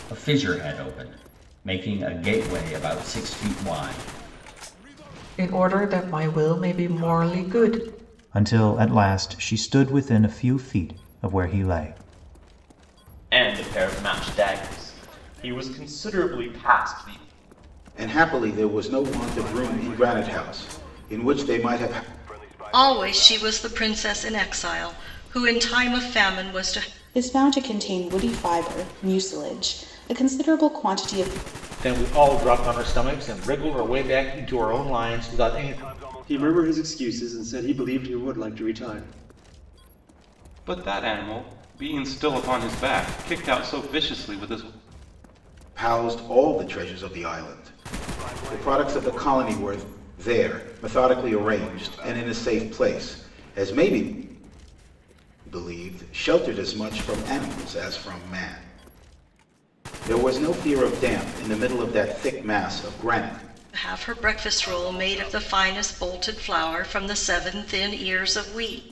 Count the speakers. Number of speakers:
10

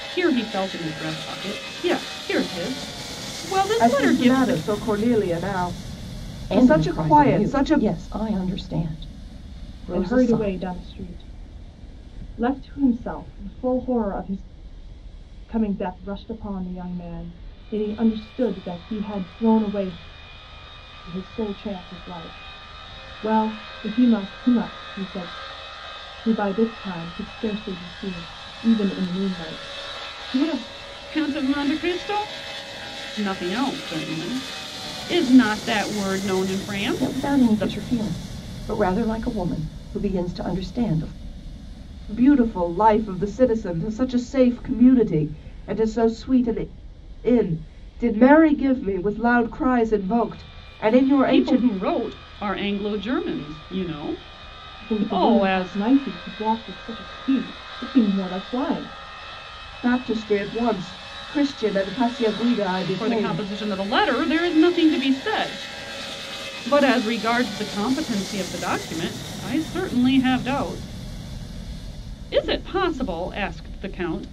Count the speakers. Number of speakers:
4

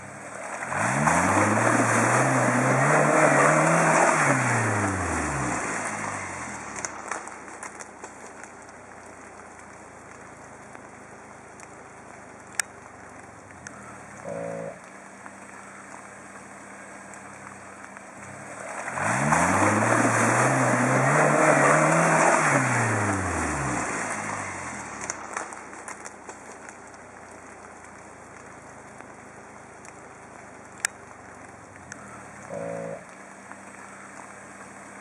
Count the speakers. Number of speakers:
0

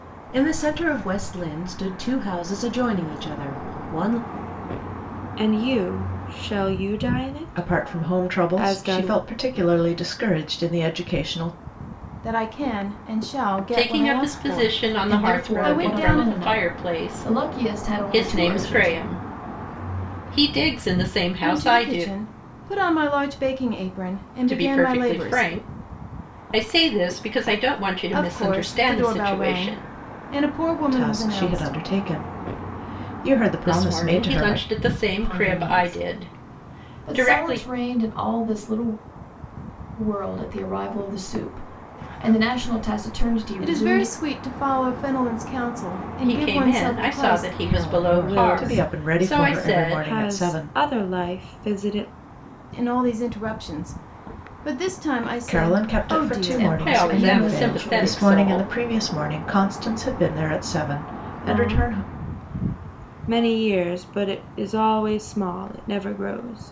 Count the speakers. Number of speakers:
6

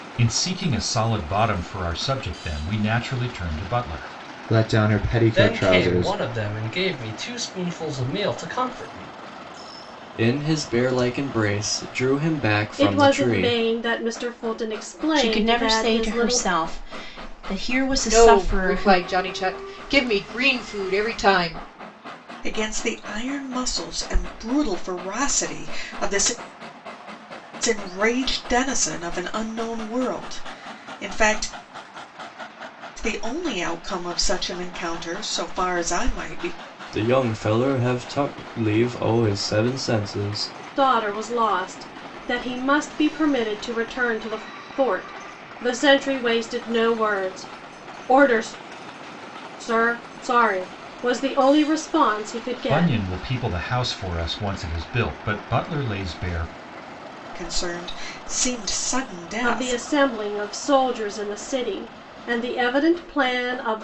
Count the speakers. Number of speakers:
8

